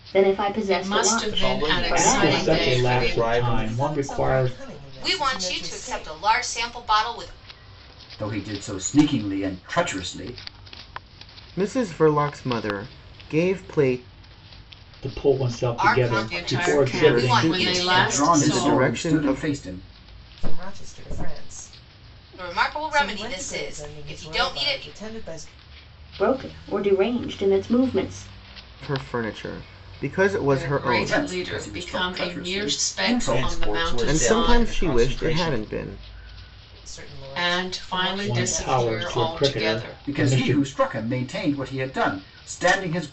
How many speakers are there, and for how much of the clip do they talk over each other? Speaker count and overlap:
eight, about 45%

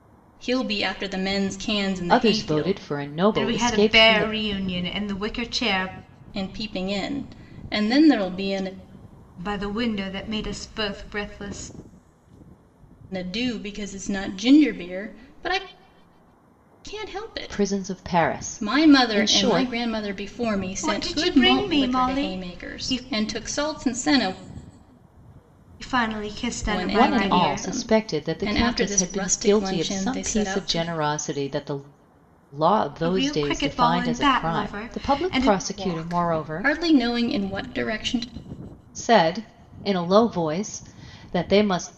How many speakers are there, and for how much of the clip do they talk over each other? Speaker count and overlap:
three, about 32%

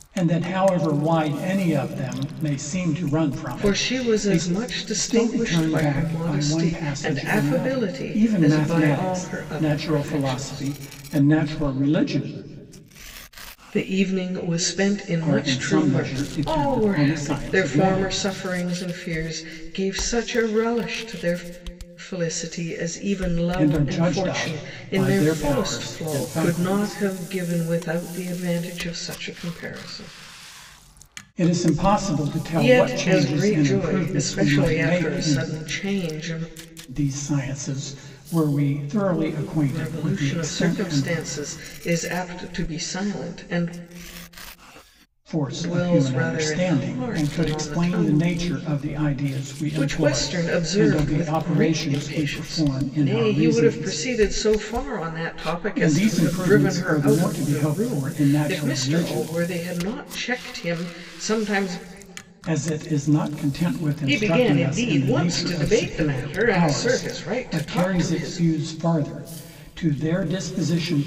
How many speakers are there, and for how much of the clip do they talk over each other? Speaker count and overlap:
two, about 45%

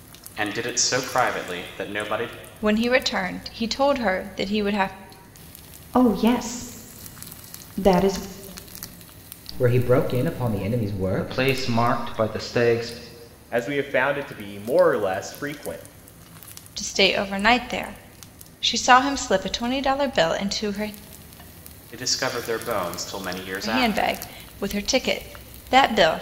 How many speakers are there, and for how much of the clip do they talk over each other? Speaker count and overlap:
six, about 3%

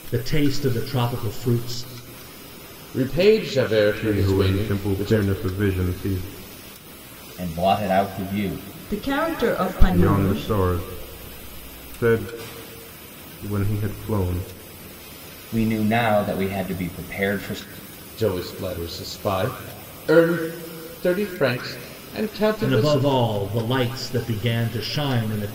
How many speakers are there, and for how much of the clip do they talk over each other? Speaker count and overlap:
five, about 9%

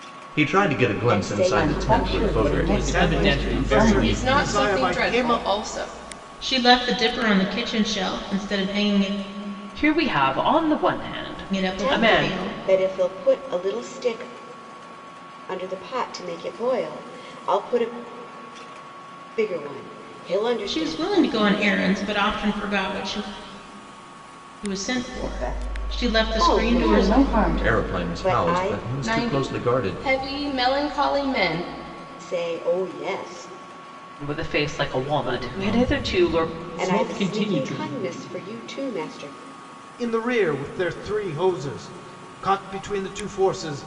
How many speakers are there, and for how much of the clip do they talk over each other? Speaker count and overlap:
eight, about 32%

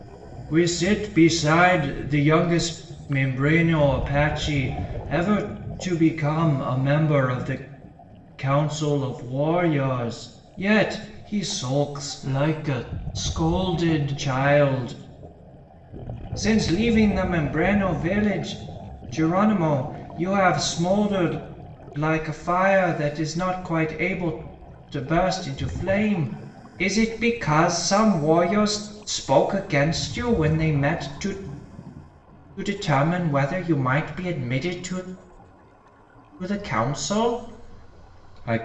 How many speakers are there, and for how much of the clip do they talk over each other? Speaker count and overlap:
one, no overlap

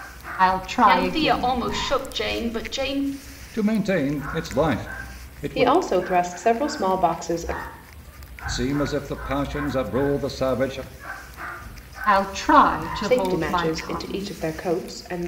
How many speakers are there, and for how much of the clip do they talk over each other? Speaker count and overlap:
four, about 15%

